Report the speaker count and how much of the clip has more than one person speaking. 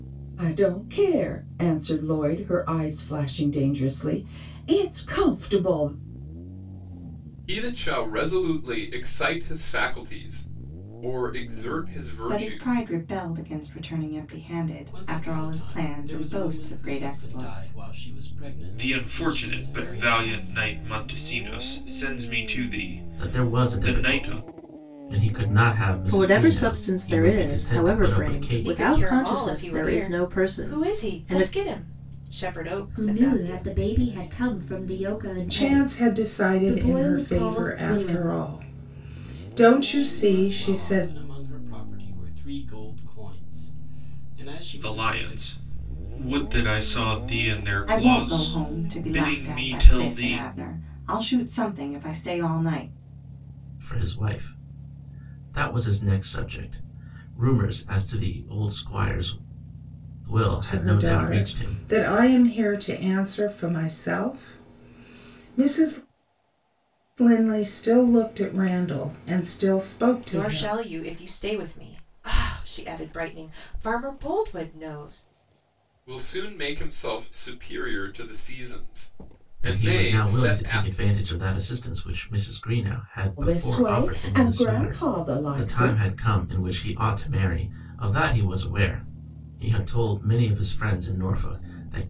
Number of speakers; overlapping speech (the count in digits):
10, about 28%